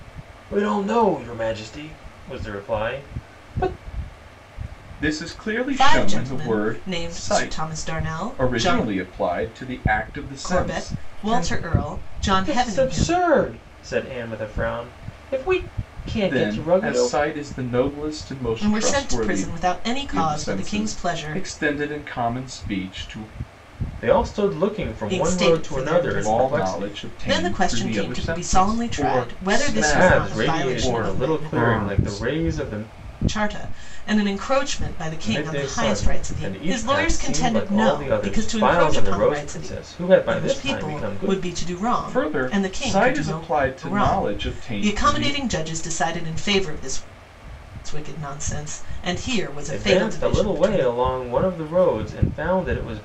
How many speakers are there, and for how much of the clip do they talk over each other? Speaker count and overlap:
3, about 46%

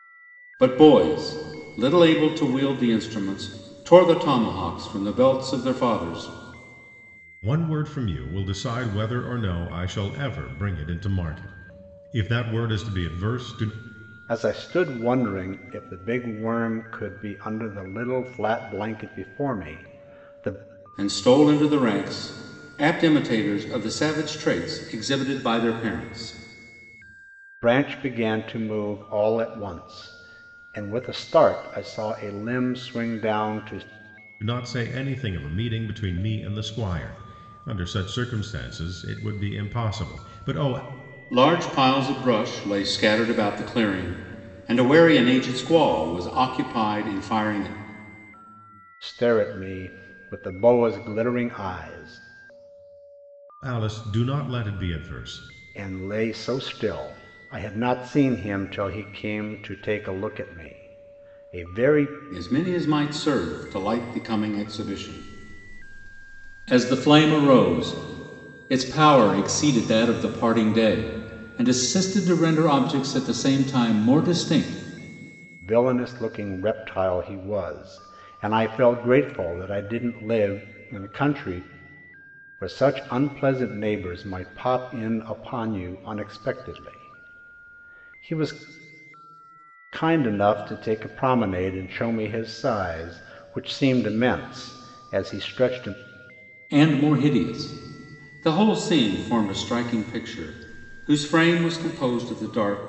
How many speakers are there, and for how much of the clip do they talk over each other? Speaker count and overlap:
3, no overlap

